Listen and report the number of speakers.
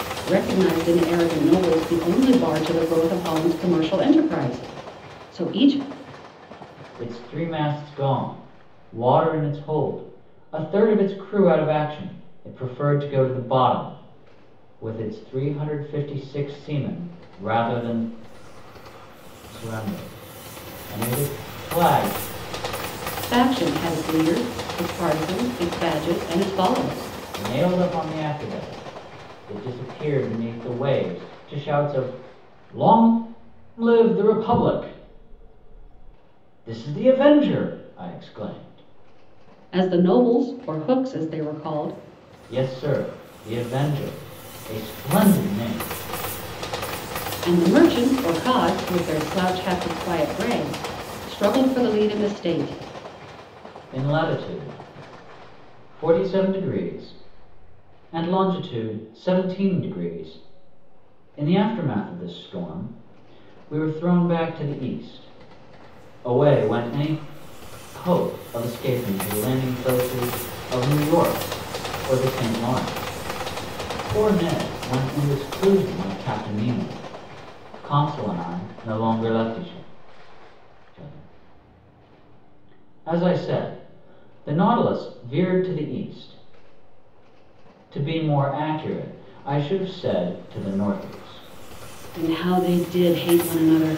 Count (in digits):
2